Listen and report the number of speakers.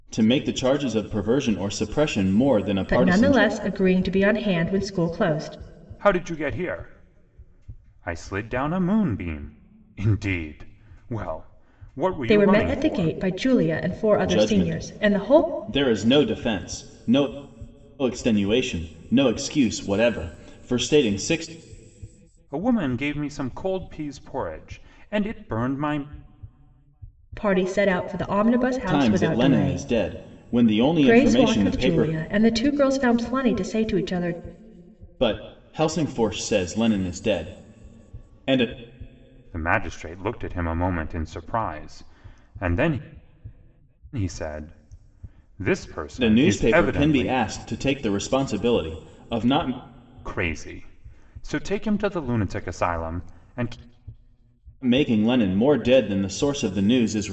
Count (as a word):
three